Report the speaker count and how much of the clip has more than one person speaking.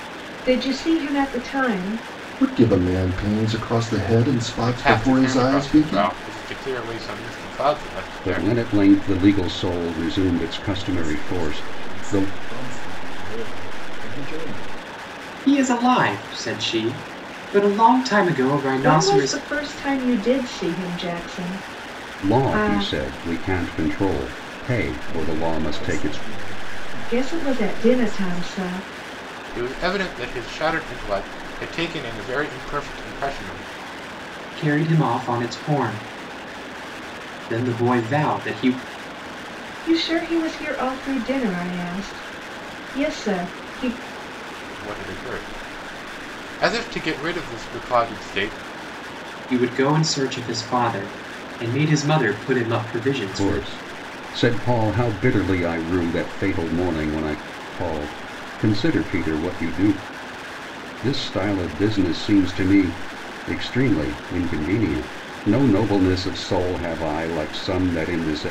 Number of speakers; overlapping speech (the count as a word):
six, about 11%